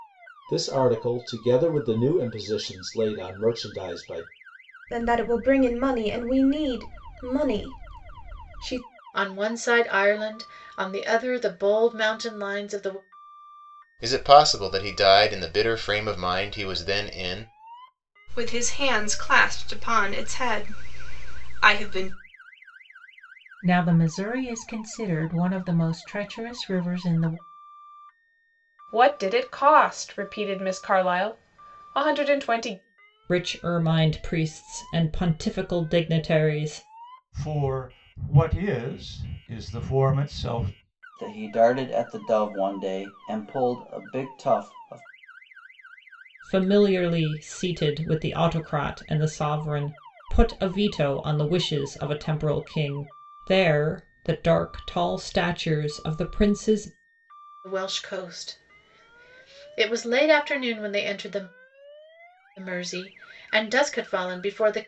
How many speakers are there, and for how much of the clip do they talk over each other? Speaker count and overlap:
10, no overlap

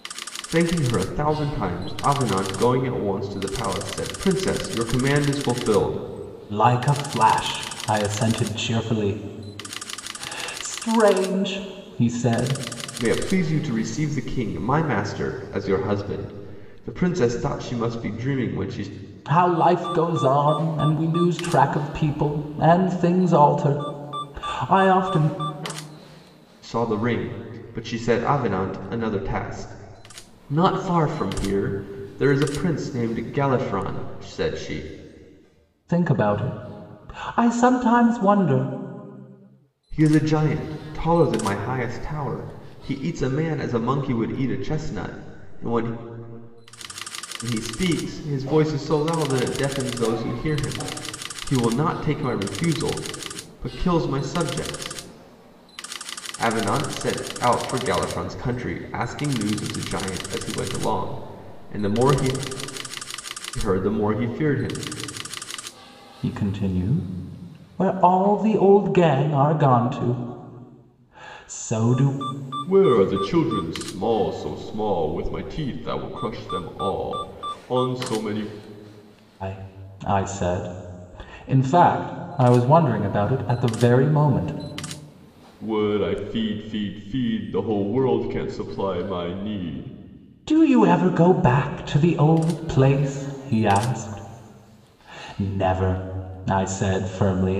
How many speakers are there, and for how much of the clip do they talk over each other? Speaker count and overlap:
2, no overlap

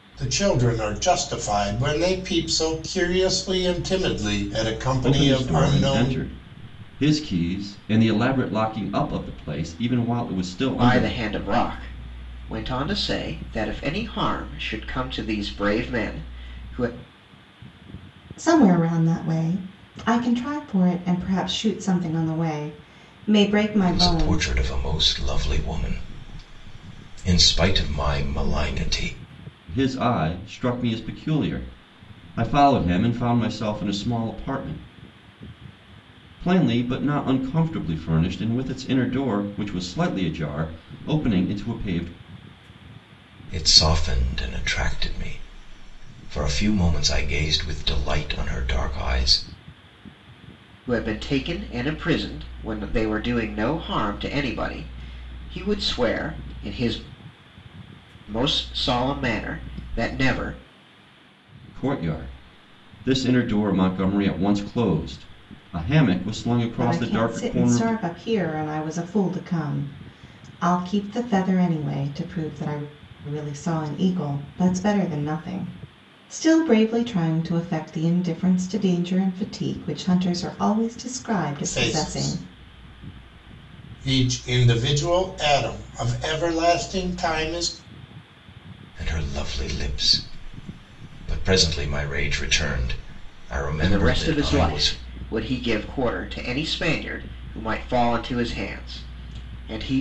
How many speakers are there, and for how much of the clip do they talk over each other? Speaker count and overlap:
5, about 6%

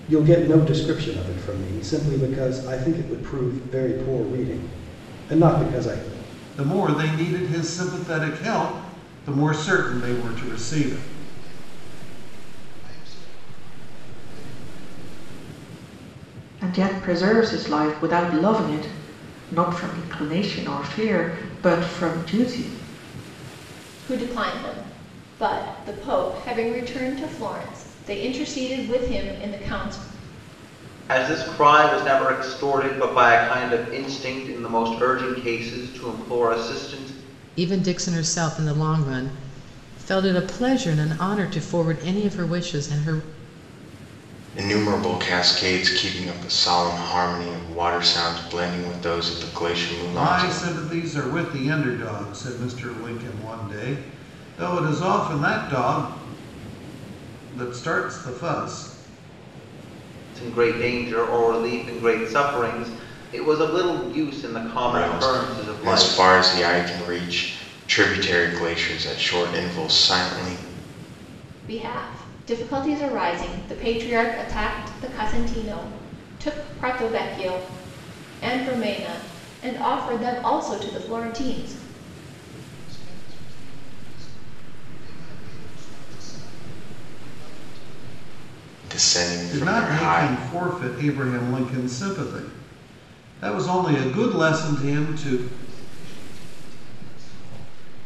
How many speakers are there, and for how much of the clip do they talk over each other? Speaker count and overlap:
8, about 6%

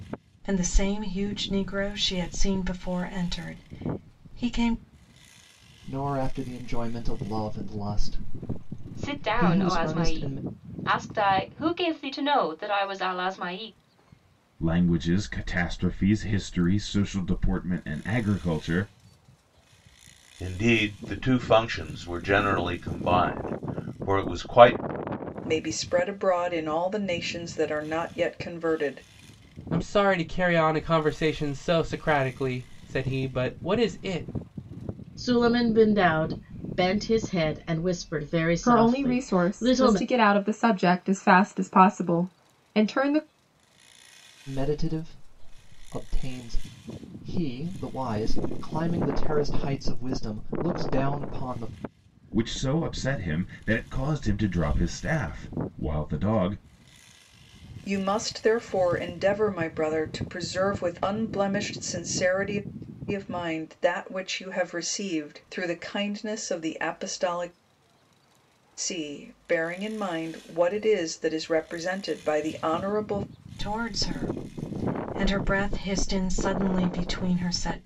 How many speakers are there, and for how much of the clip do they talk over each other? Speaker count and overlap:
9, about 4%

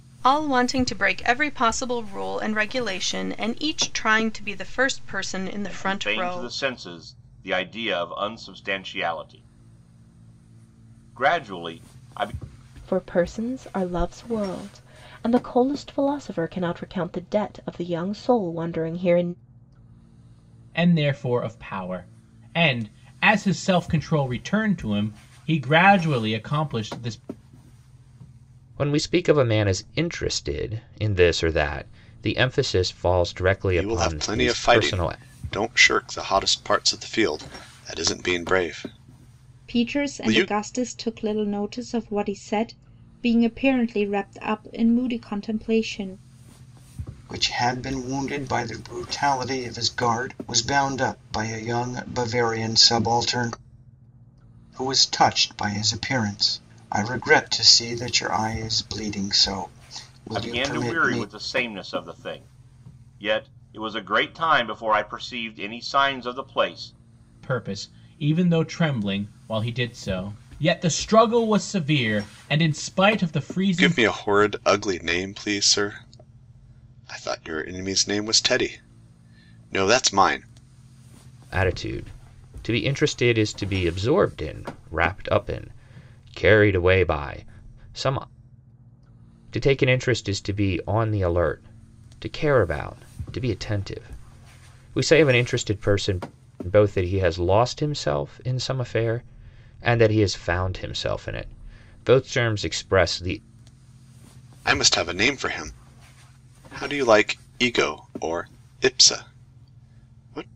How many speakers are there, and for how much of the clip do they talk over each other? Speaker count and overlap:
8, about 4%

